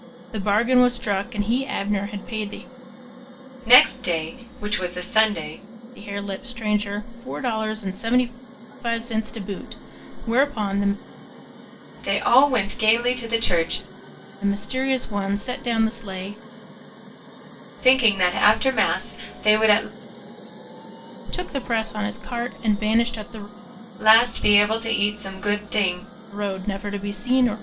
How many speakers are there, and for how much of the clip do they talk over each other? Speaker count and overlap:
two, no overlap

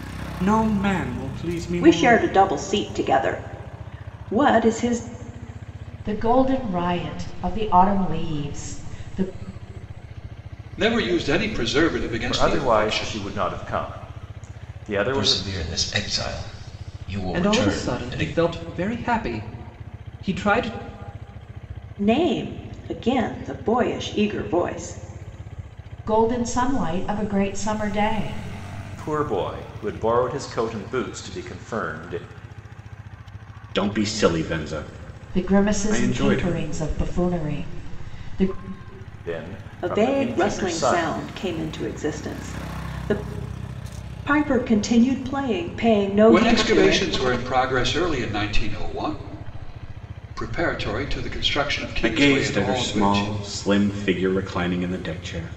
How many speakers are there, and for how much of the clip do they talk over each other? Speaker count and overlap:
seven, about 14%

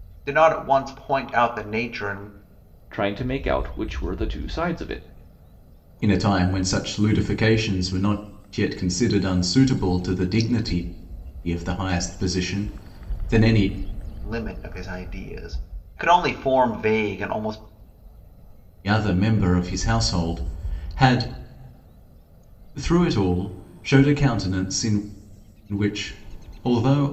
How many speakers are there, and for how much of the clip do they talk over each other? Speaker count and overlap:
three, no overlap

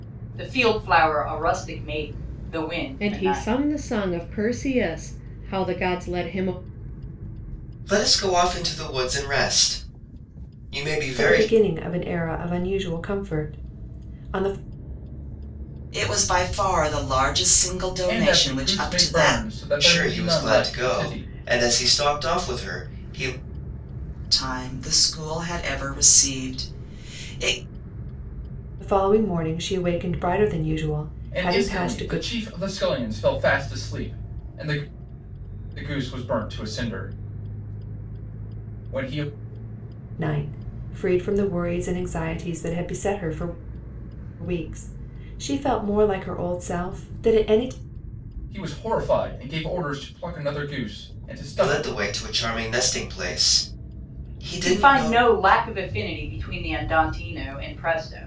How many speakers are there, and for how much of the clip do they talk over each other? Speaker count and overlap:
six, about 10%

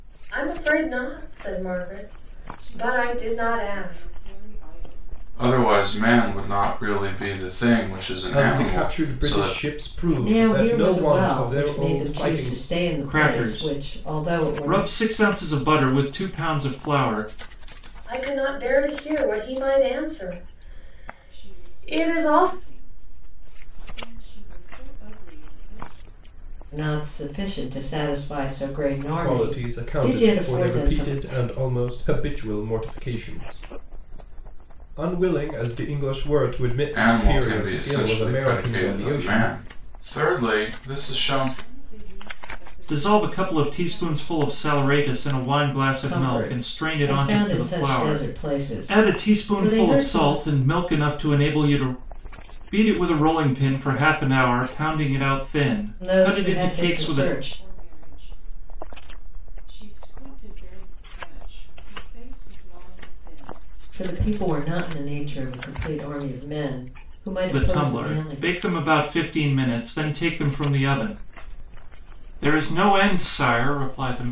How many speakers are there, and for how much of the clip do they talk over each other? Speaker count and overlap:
six, about 36%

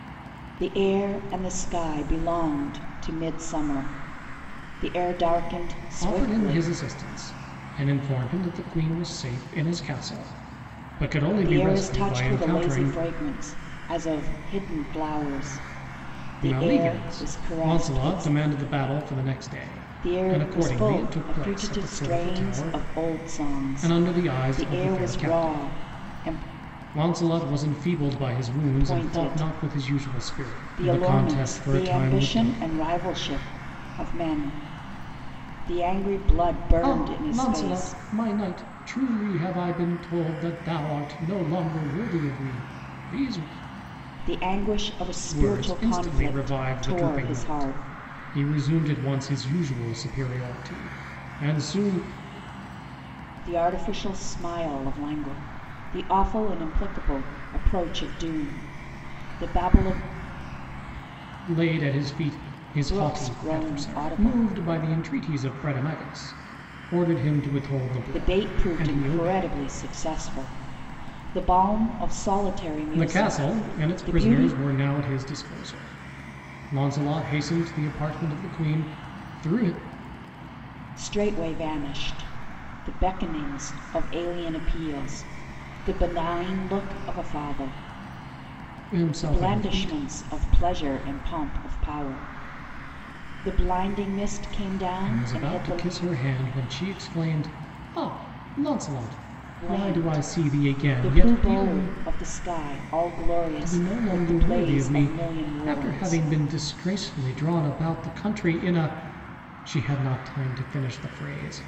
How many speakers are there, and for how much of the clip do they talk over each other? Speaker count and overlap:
two, about 26%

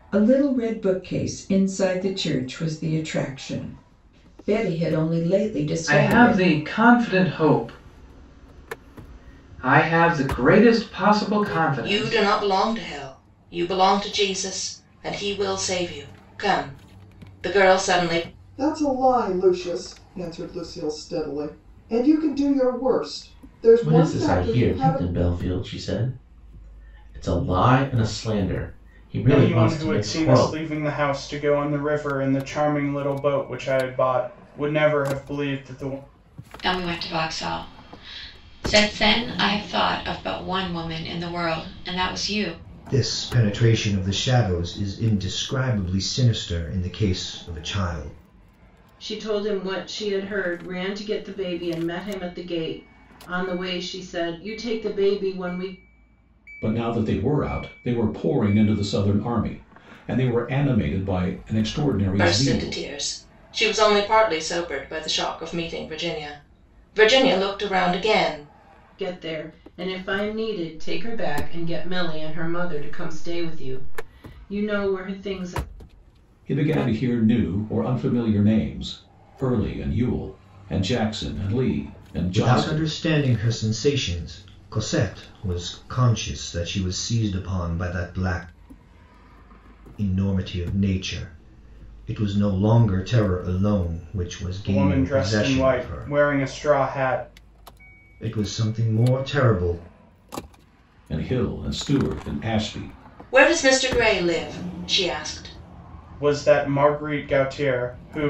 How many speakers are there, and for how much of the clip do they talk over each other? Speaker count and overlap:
ten, about 6%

